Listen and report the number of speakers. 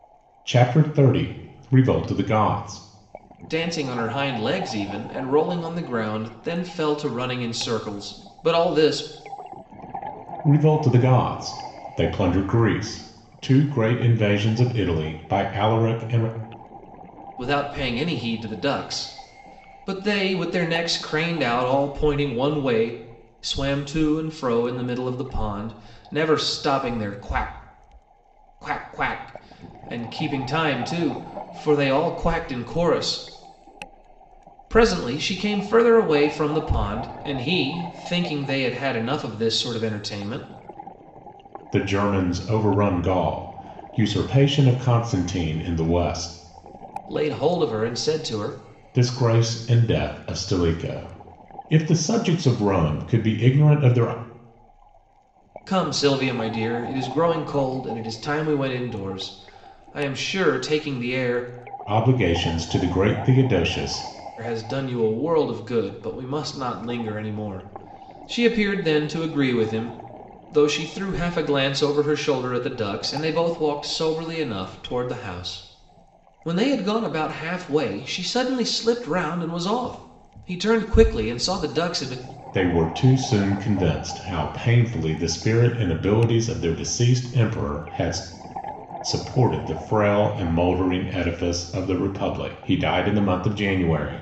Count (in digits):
2